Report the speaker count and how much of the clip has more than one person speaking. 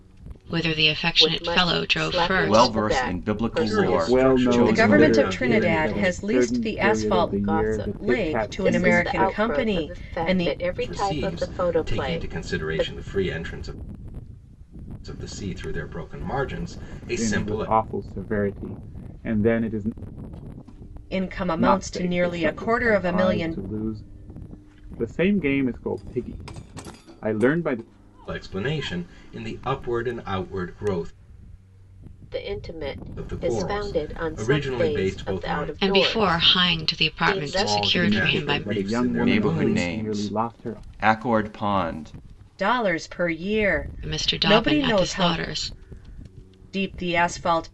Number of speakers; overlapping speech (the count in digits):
6, about 49%